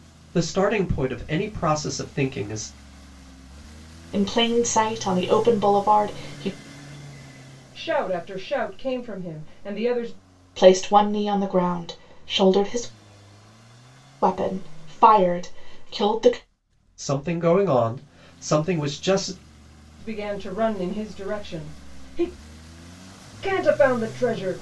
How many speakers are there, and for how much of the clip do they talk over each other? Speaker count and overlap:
three, no overlap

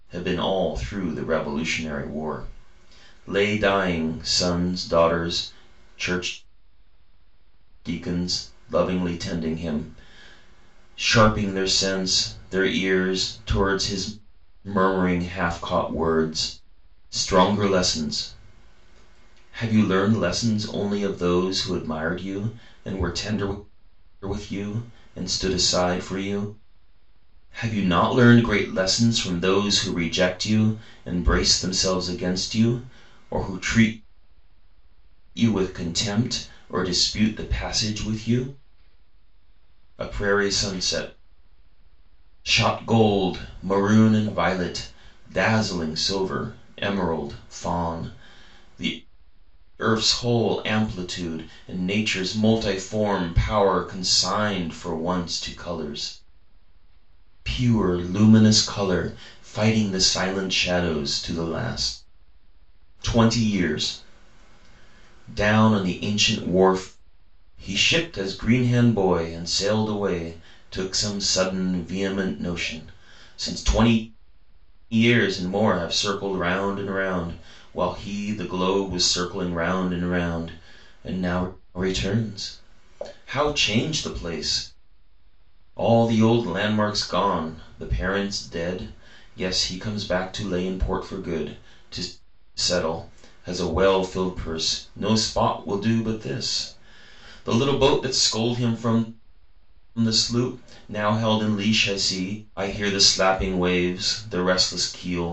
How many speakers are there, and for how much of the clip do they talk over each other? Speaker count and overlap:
one, no overlap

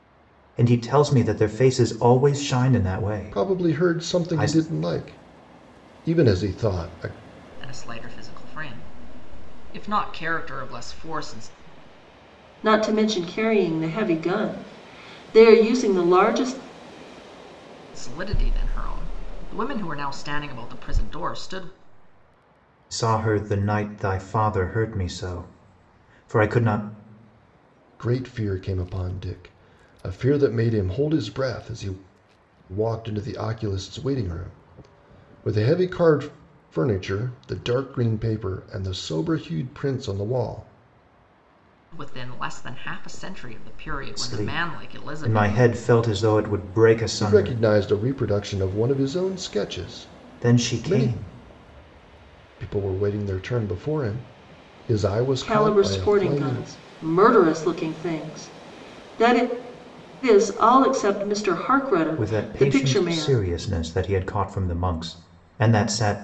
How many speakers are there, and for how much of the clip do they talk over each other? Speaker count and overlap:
four, about 10%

